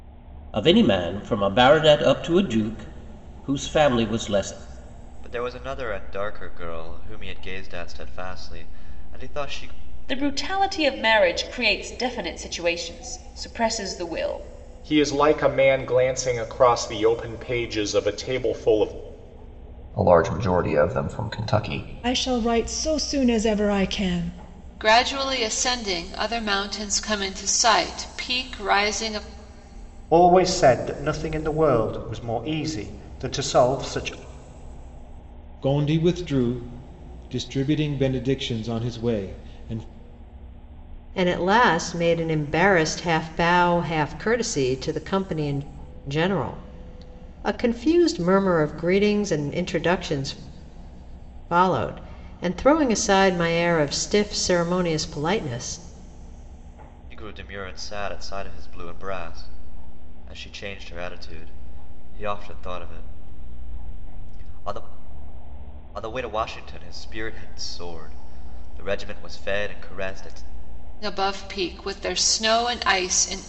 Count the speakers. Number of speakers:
10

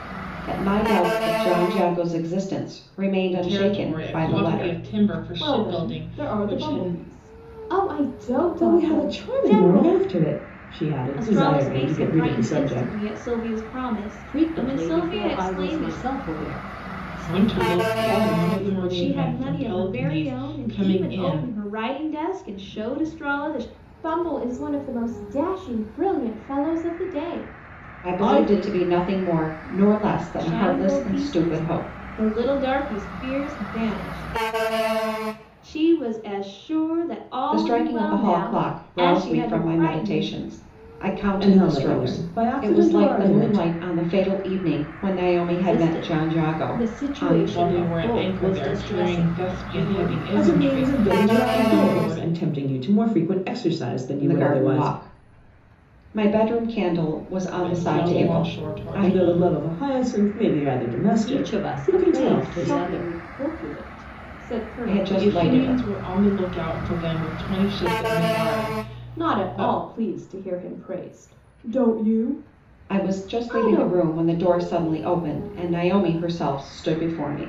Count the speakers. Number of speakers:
6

